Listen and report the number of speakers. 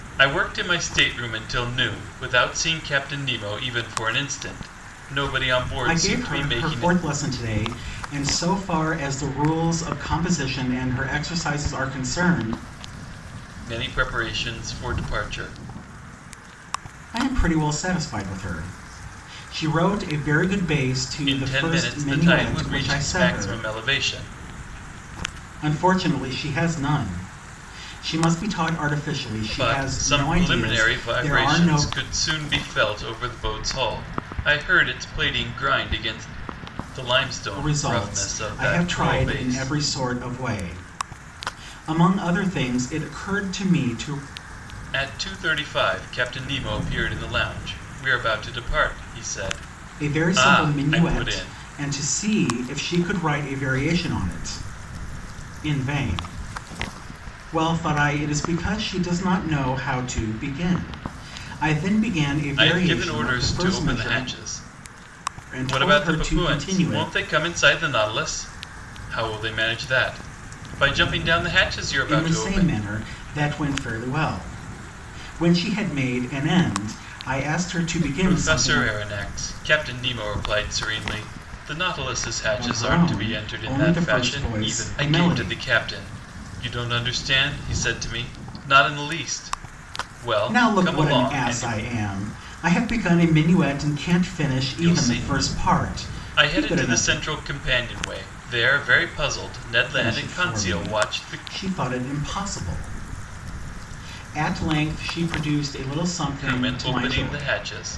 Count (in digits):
2